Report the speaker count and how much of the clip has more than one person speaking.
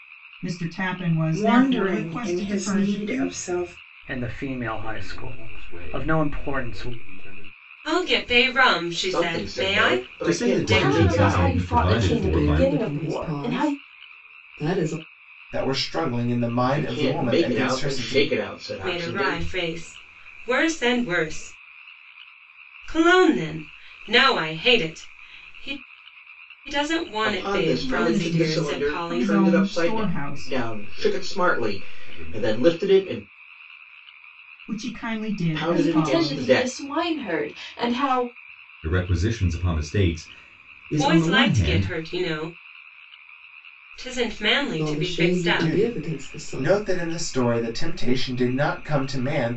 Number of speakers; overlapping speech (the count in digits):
10, about 43%